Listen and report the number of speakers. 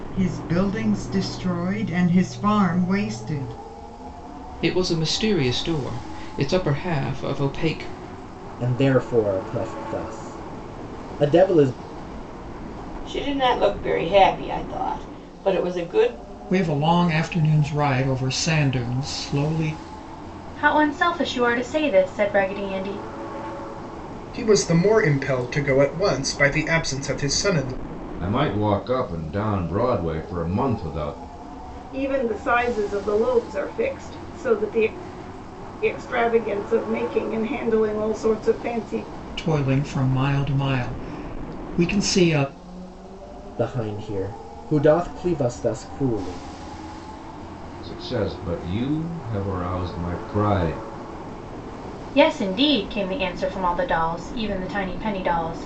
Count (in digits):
9